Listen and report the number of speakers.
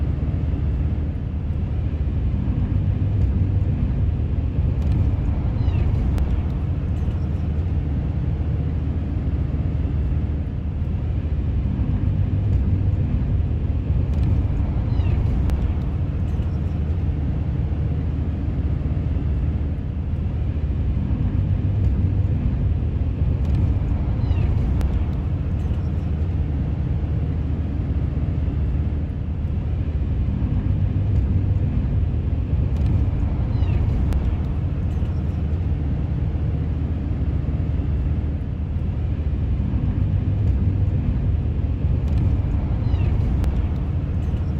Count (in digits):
0